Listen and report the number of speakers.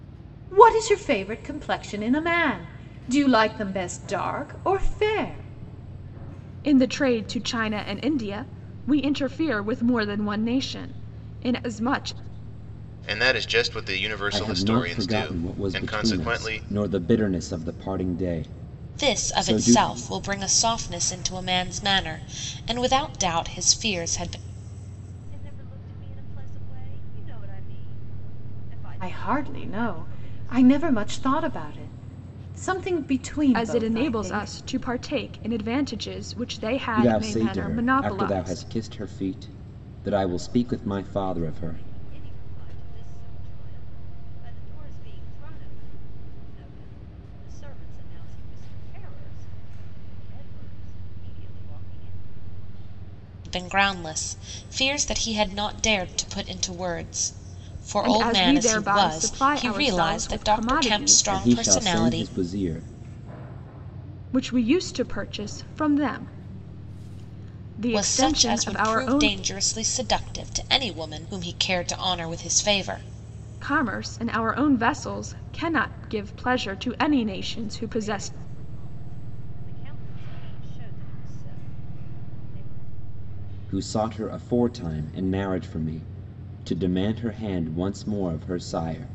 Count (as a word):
six